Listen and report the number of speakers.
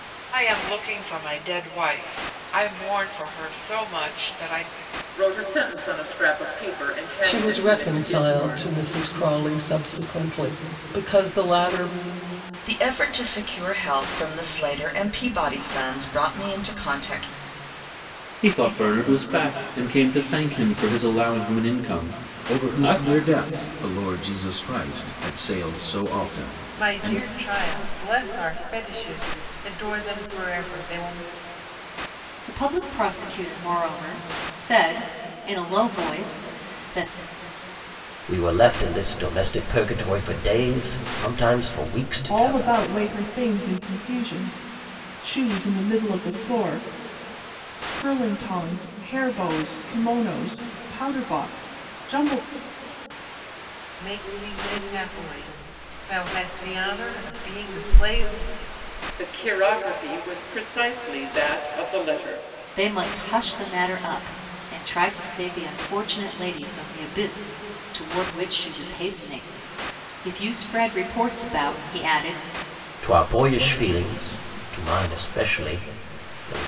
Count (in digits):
10